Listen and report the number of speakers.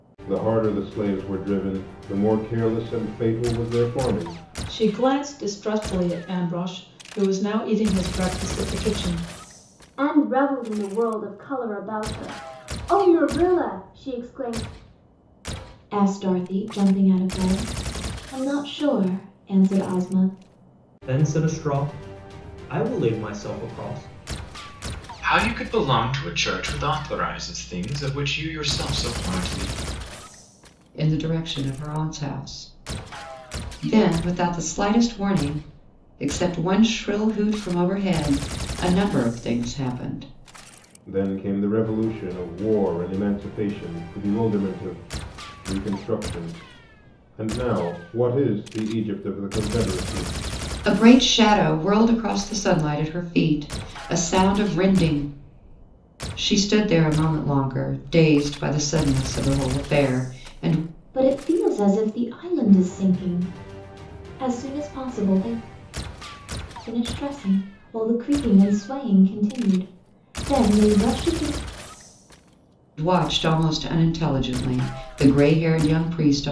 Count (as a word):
seven